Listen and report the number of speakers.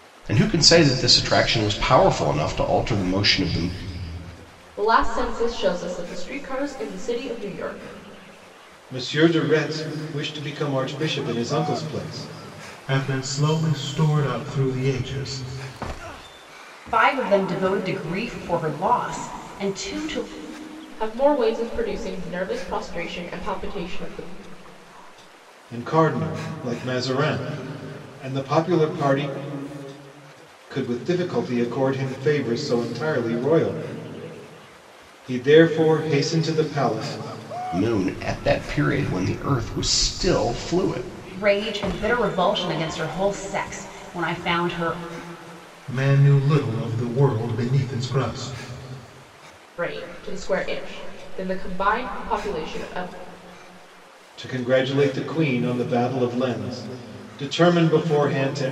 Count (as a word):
five